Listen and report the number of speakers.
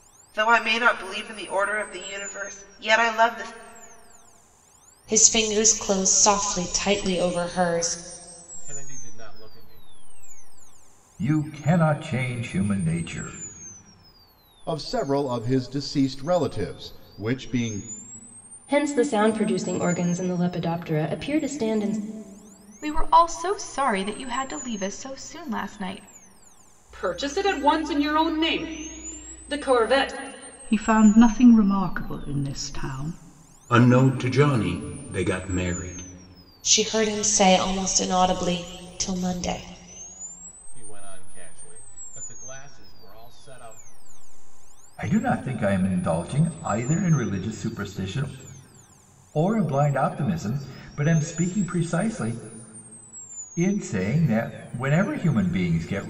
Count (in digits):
10